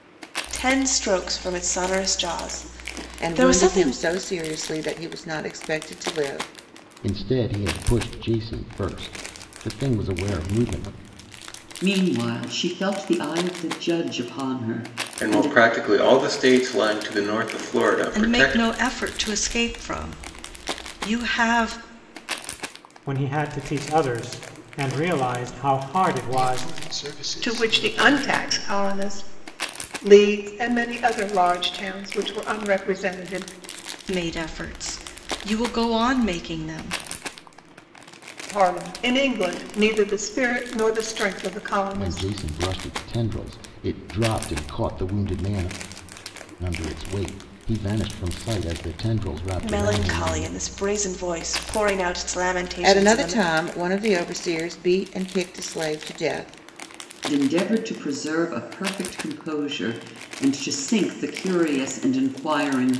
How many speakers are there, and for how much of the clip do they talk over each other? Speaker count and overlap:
nine, about 9%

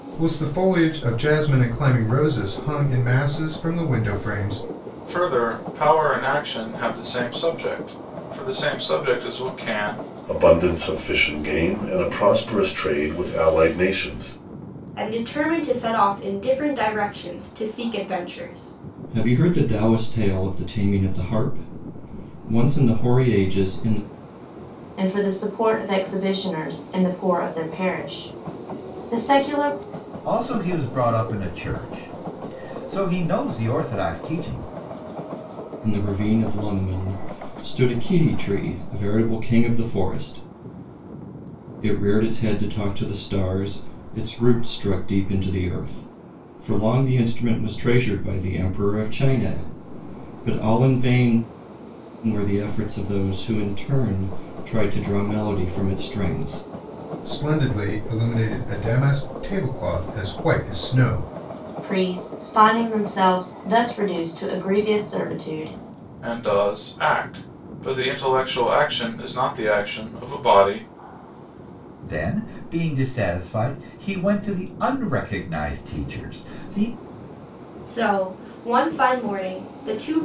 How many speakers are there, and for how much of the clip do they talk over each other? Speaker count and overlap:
seven, no overlap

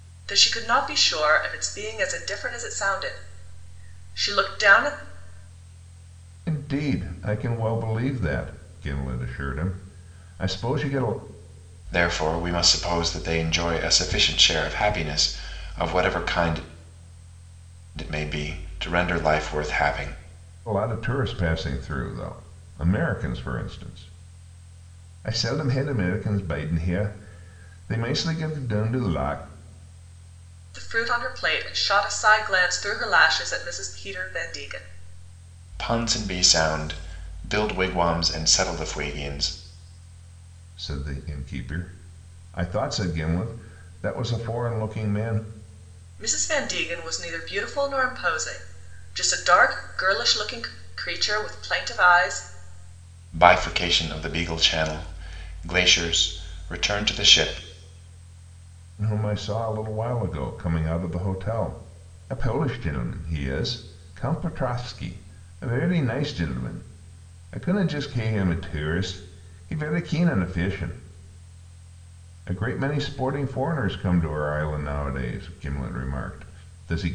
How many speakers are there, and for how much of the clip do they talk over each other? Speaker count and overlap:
three, no overlap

